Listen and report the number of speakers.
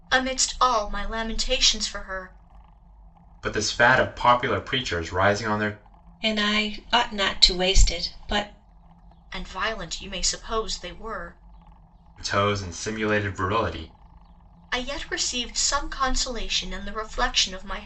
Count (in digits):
3